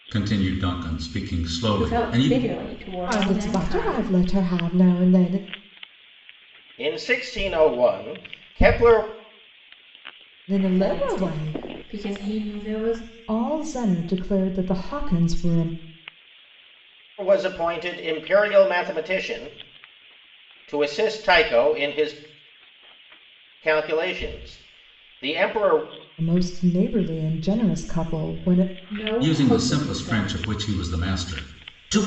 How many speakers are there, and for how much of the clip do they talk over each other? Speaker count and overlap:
4, about 12%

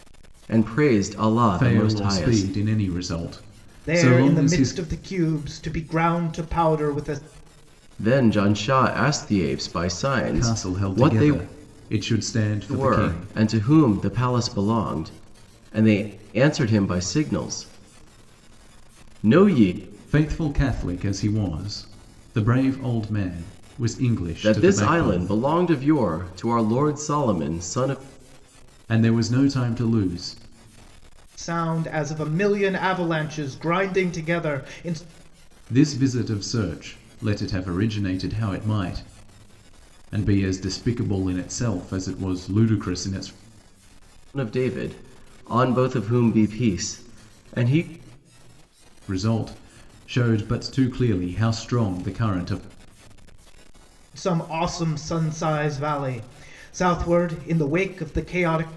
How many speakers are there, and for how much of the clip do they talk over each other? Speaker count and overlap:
3, about 8%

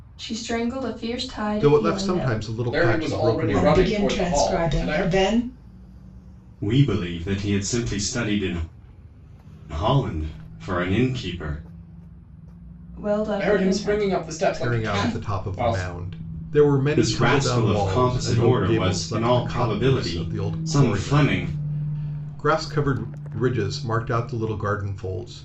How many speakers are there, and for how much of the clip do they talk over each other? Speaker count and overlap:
5, about 41%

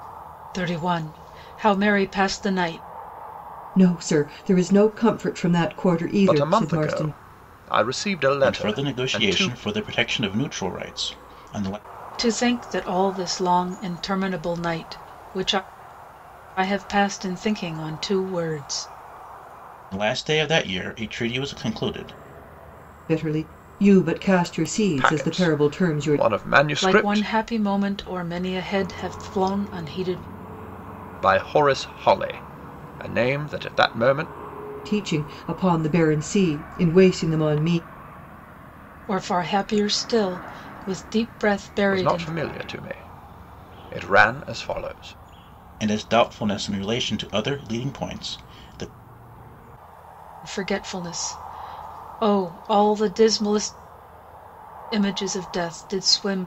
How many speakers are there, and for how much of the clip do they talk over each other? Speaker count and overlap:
4, about 8%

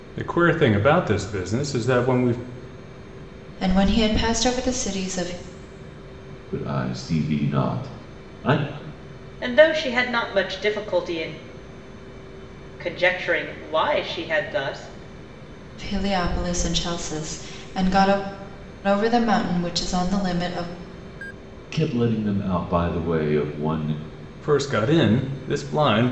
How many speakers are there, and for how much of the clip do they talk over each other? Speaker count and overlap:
4, no overlap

